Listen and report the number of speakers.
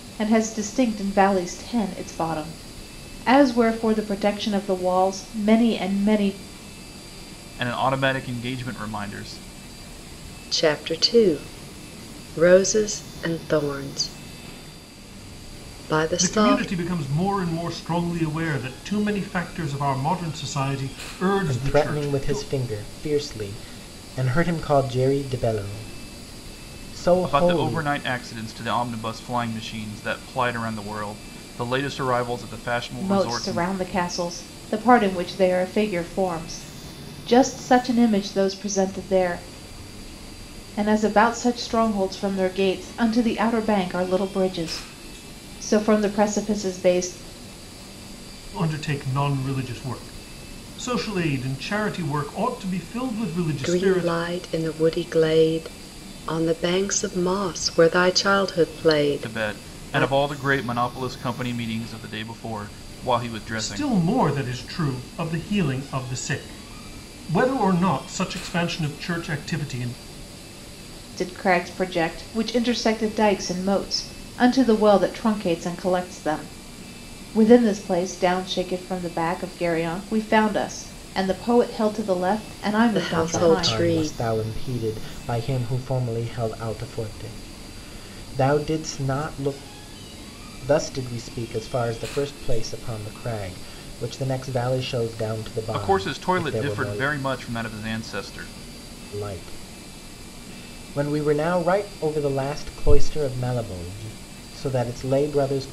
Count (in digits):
5